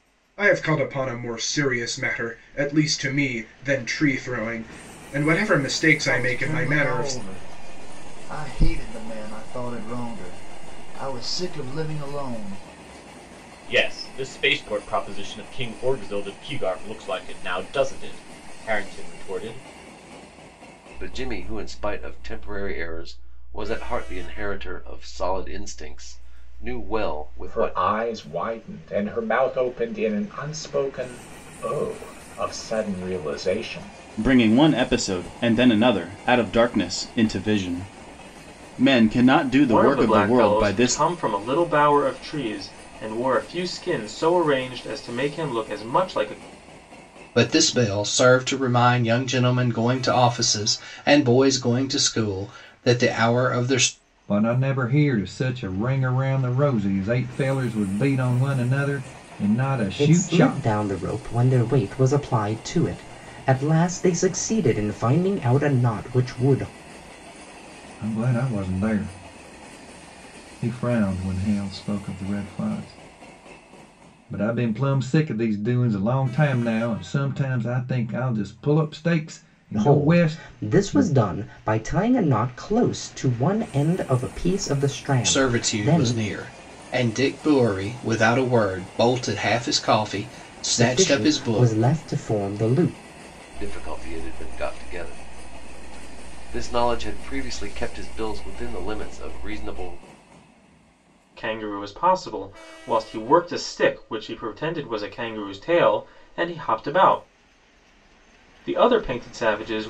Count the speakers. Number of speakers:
ten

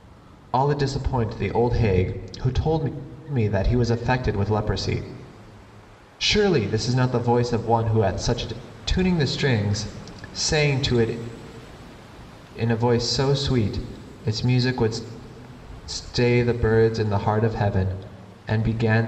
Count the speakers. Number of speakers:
one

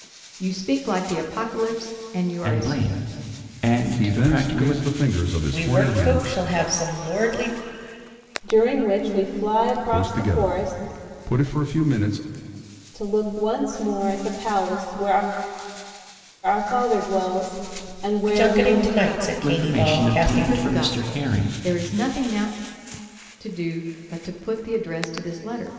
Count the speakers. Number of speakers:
five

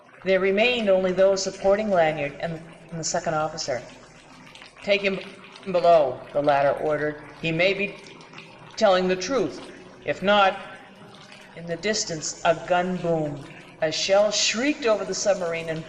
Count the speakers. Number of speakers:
one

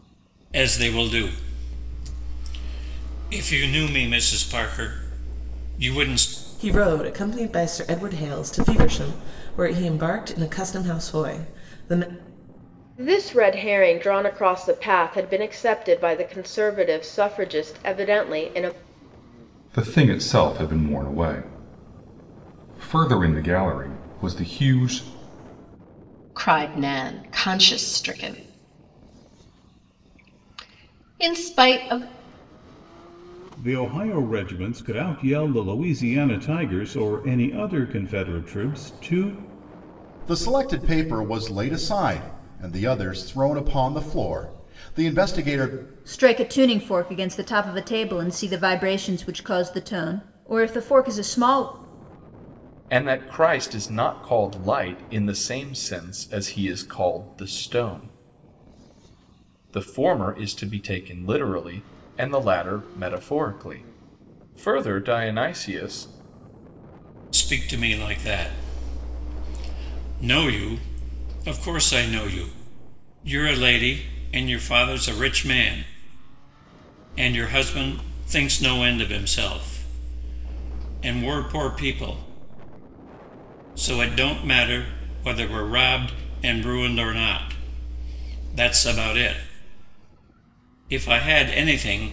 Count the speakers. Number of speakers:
nine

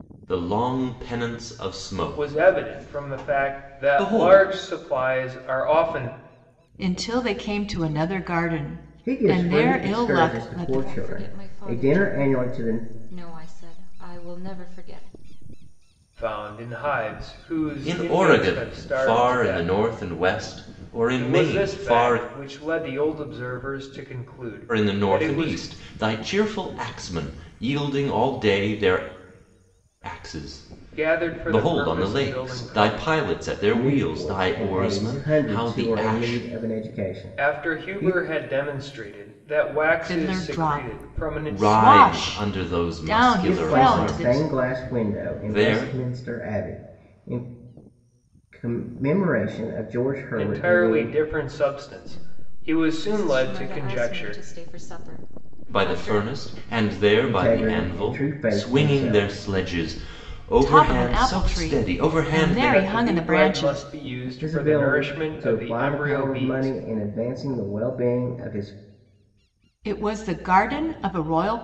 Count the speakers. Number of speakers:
five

